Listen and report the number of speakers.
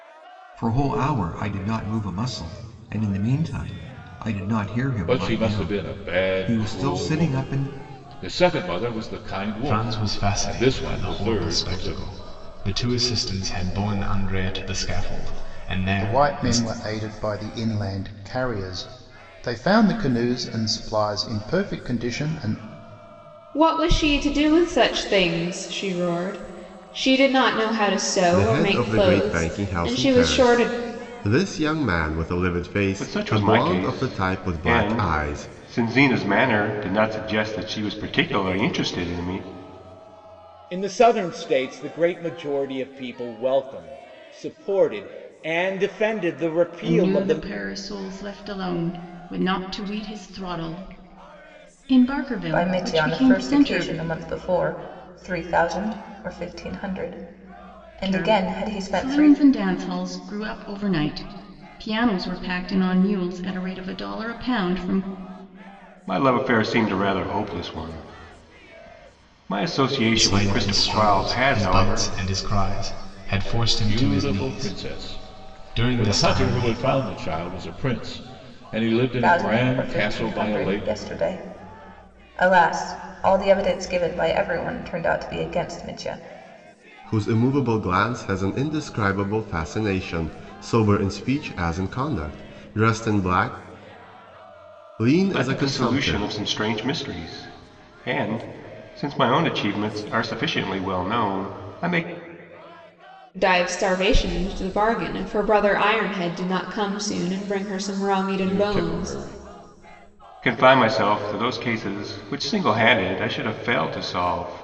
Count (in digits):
10